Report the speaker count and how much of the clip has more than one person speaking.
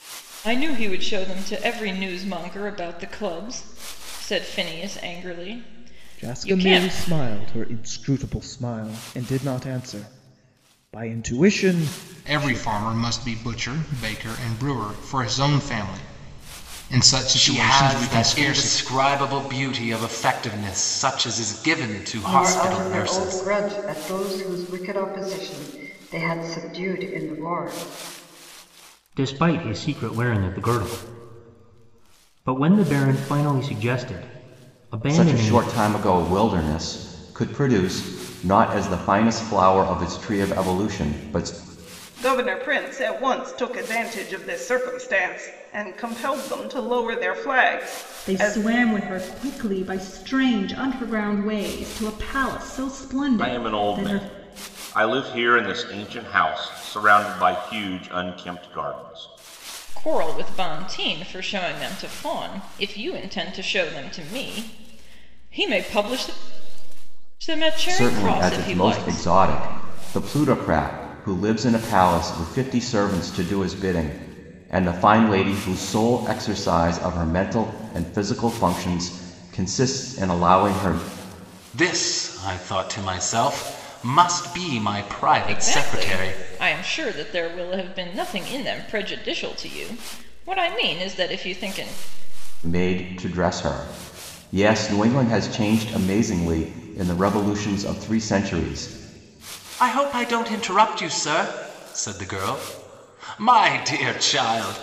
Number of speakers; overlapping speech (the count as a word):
ten, about 8%